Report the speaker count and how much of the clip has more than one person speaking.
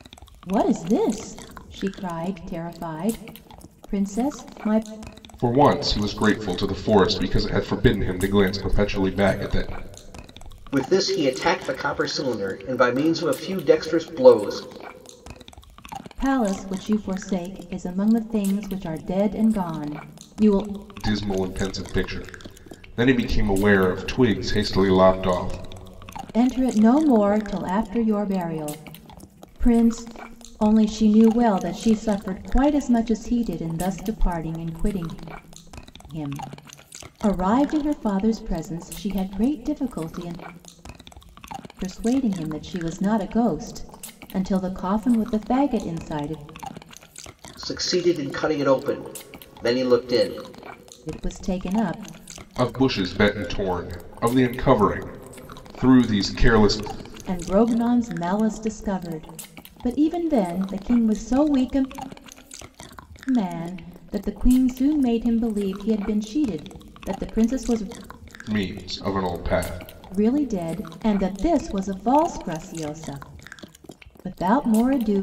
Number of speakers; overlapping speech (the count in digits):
3, no overlap